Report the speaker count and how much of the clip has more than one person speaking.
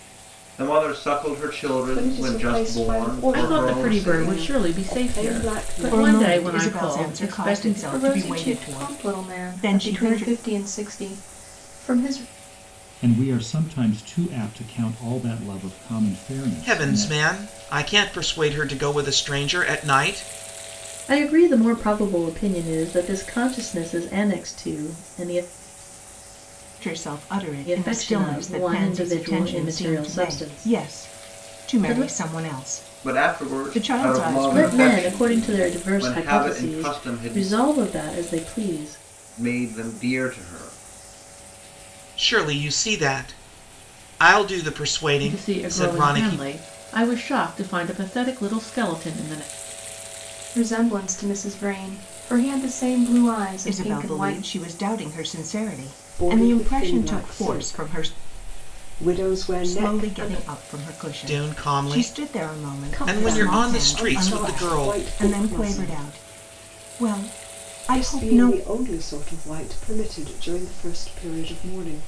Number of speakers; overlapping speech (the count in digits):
8, about 39%